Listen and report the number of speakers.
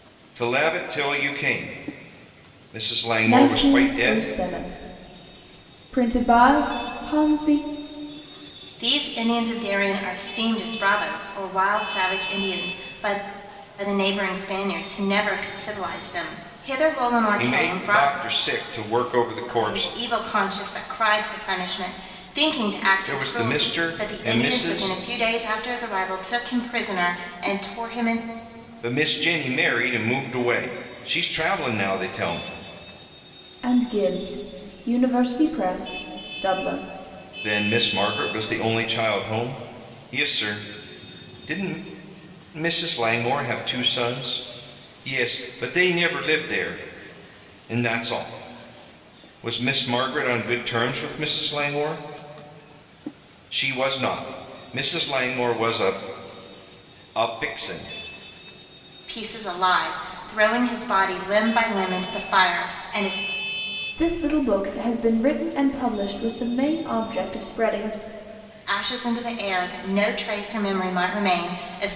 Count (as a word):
three